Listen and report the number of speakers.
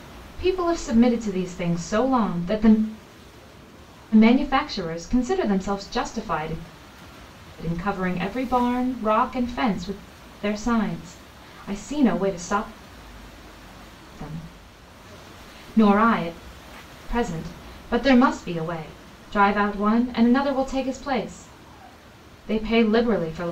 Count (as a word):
one